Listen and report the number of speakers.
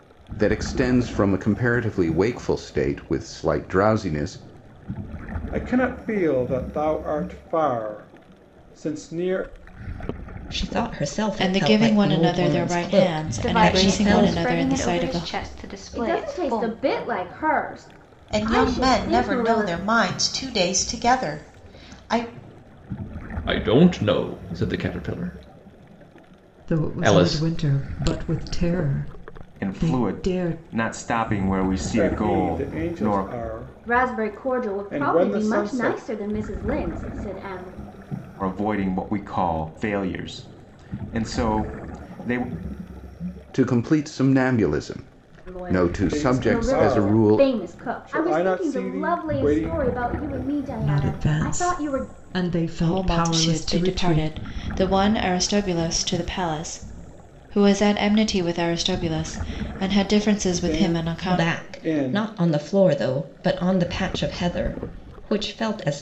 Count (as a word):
ten